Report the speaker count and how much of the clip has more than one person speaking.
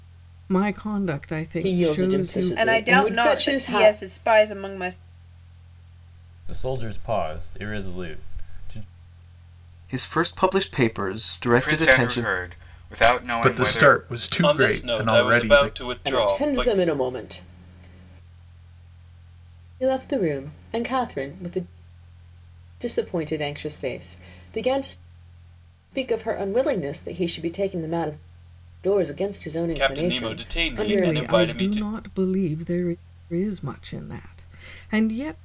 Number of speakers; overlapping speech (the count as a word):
eight, about 23%